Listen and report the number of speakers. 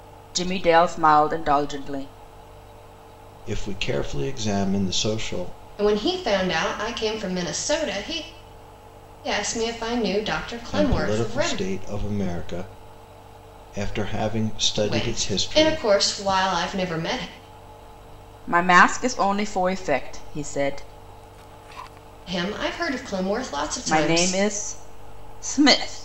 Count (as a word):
three